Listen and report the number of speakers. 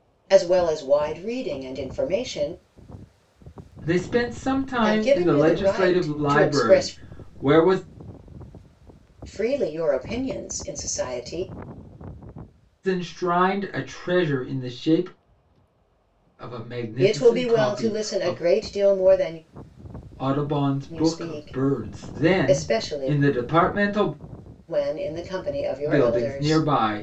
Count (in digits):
2